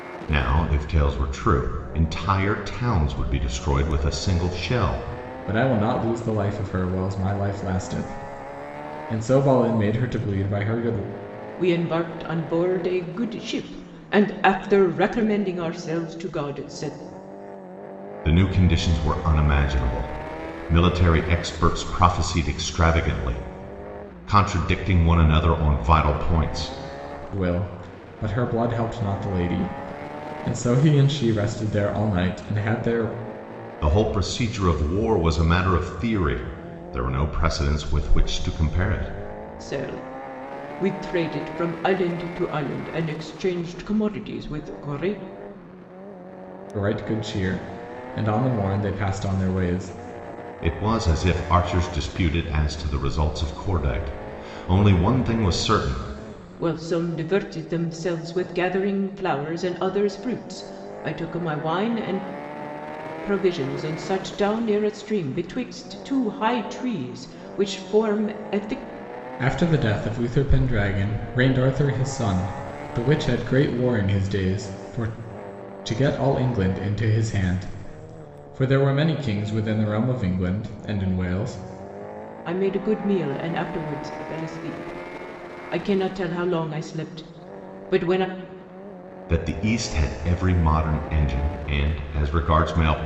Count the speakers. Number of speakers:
3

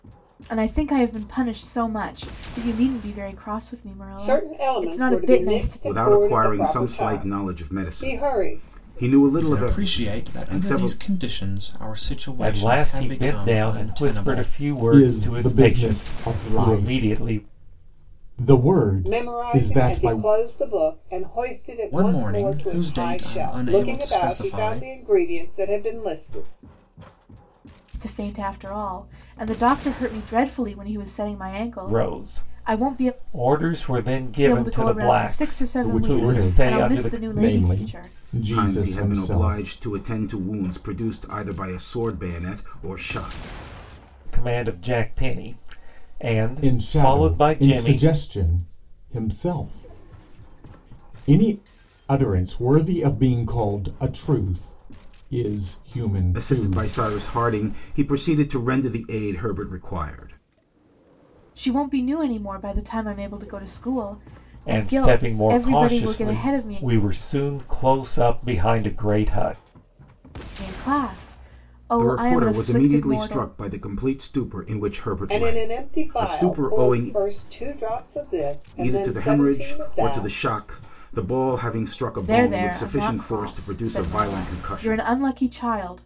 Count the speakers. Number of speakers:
6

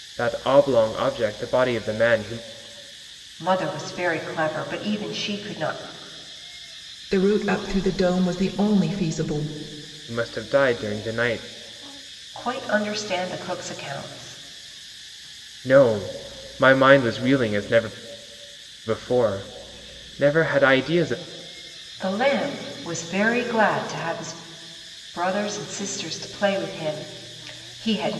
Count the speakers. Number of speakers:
3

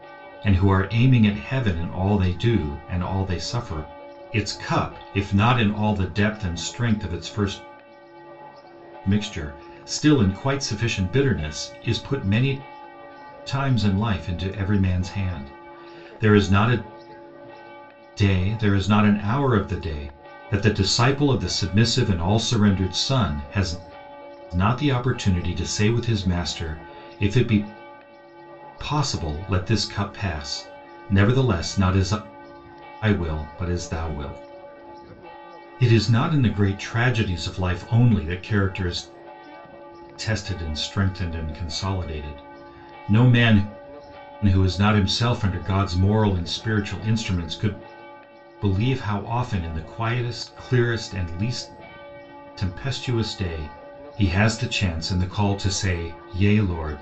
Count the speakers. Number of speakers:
1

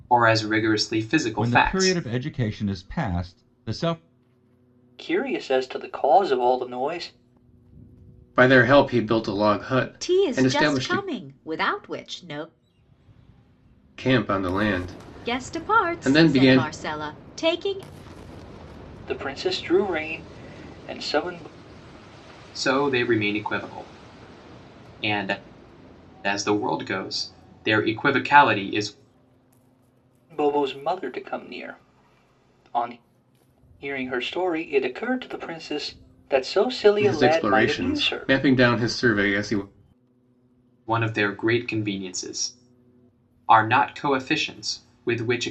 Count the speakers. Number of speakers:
5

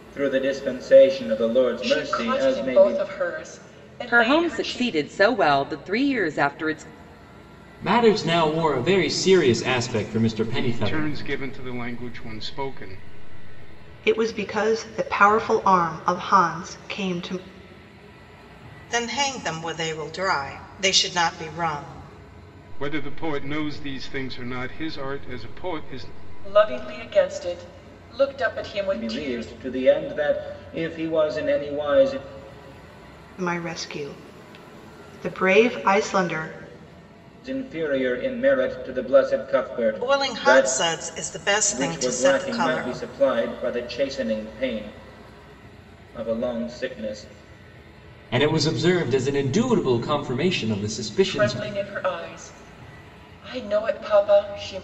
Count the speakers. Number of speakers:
7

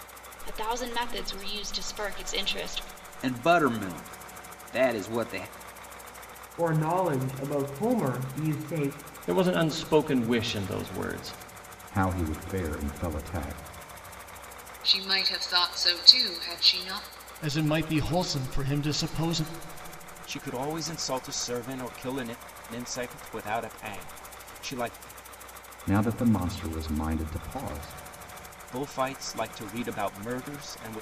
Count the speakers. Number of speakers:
8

